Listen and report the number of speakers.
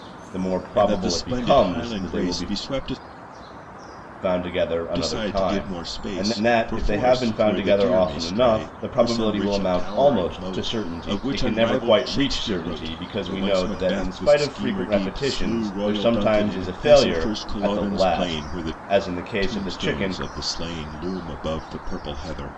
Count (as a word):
two